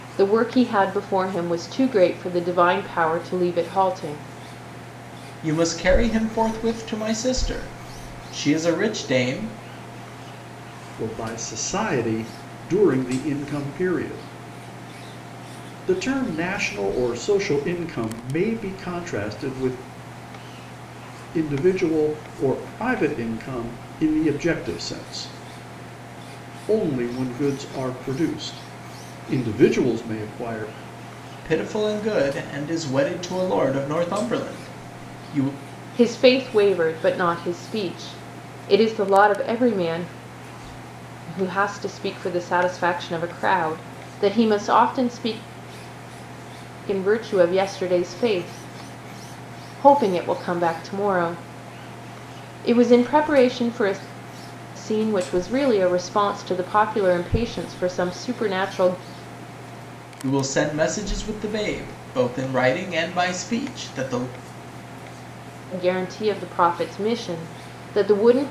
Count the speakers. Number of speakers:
three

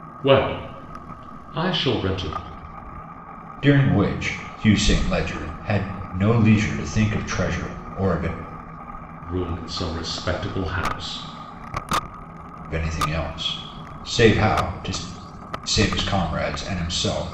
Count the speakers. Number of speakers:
two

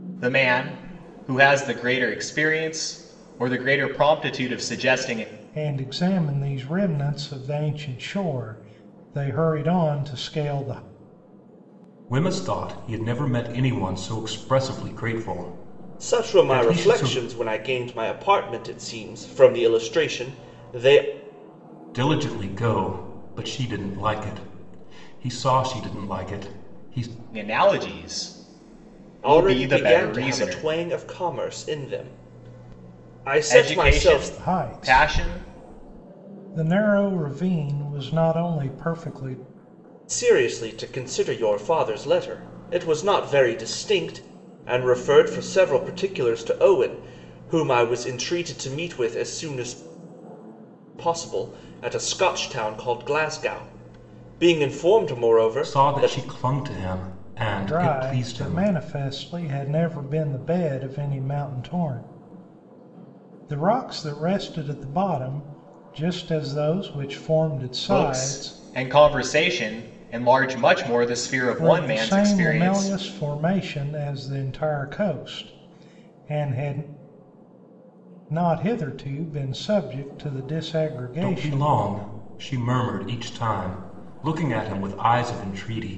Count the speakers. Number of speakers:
four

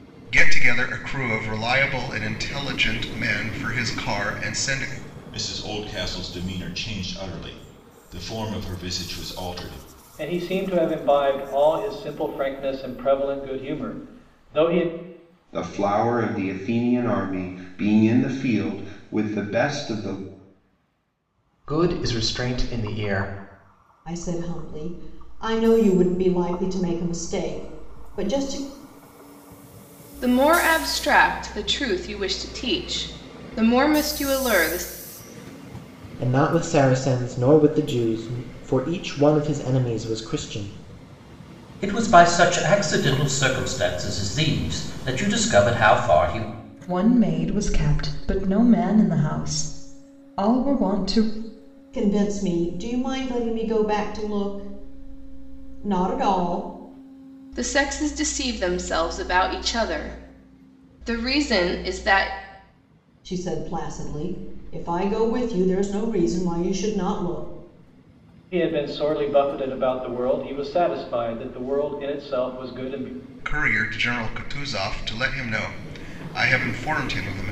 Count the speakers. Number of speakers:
ten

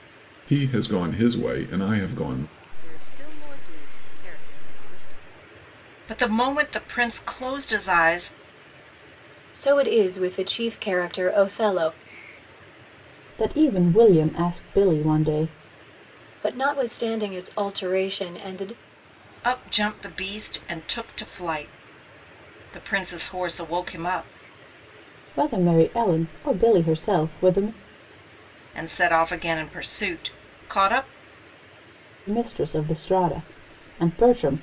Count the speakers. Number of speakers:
five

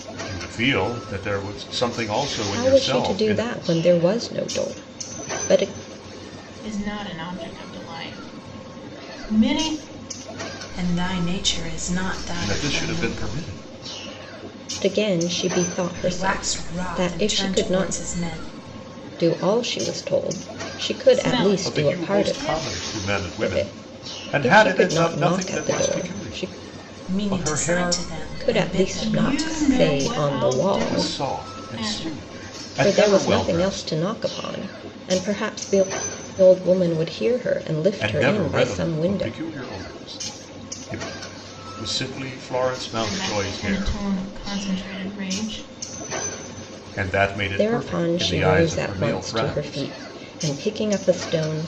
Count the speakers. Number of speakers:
four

